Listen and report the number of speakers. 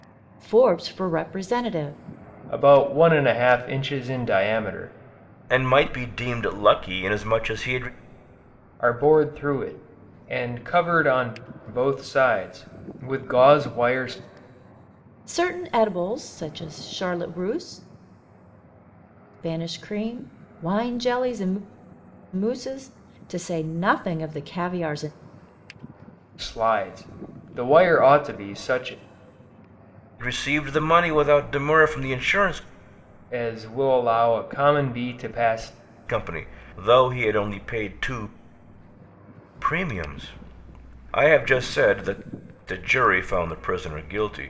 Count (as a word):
three